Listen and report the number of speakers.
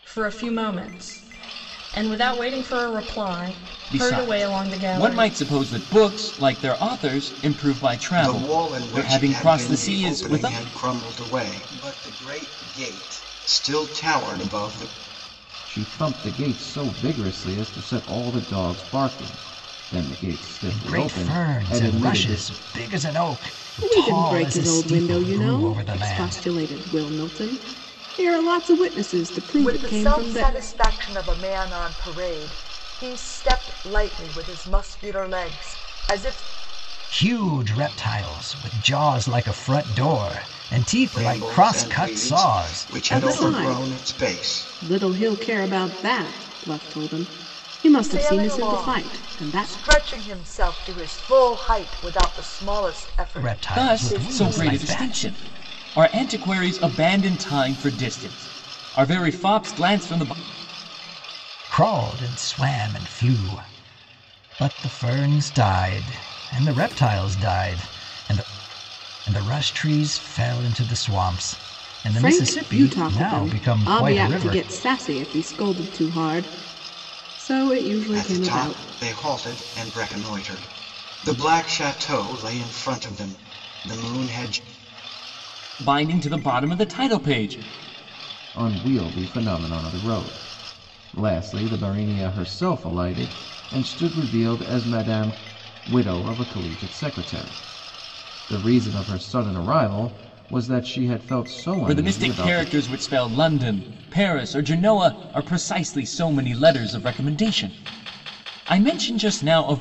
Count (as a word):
seven